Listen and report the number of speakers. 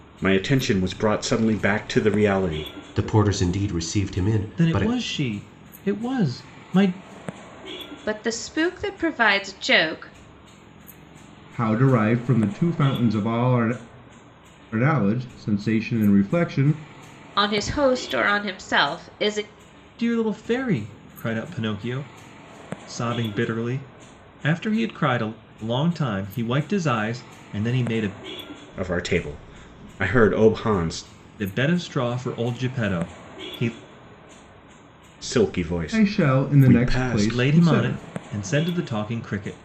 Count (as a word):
five